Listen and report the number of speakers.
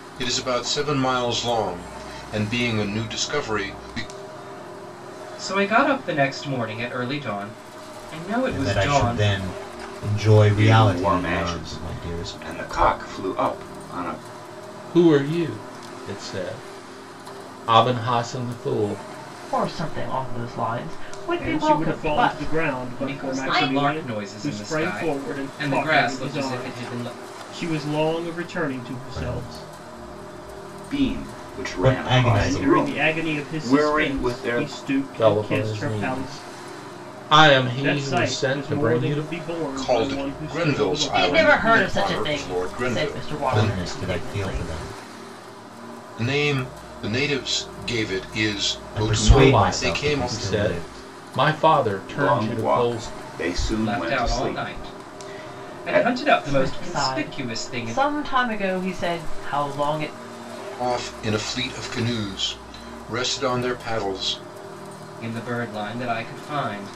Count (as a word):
seven